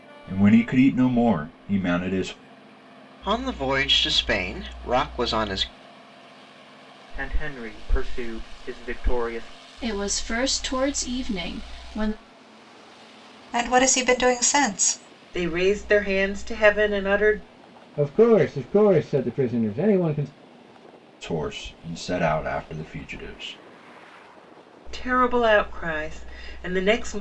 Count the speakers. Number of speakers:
7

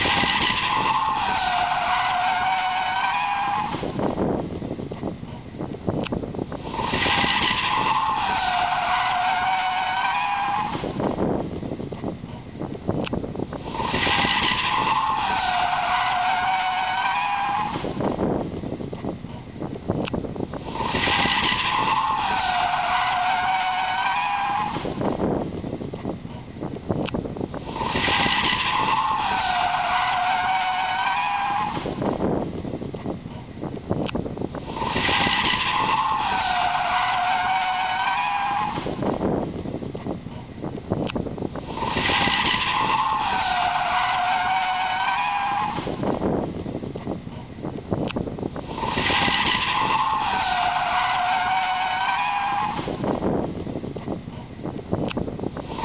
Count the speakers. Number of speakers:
0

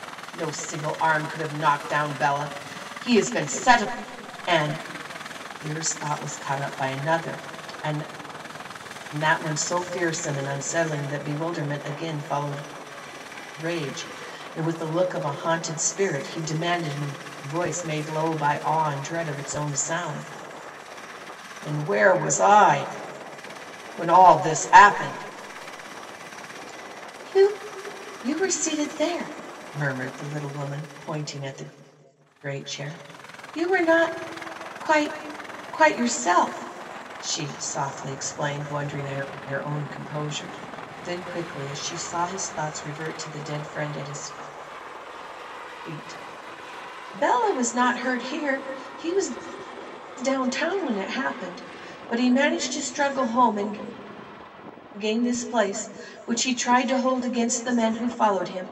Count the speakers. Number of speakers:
1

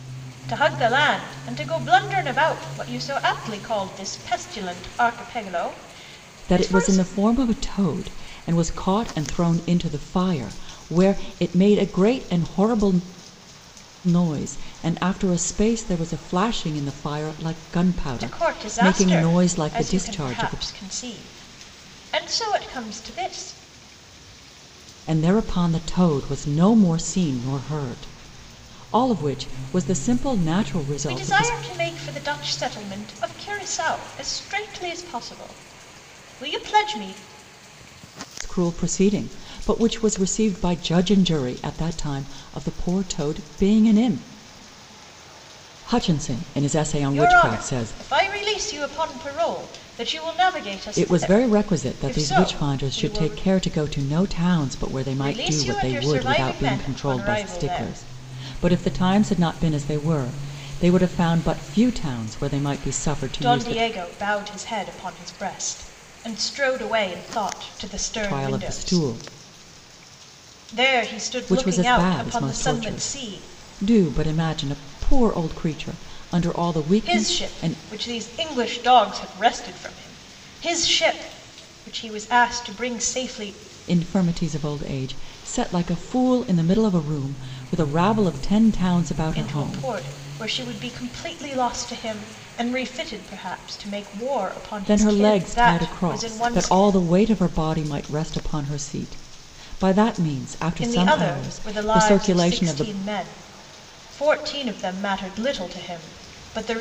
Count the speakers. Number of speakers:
2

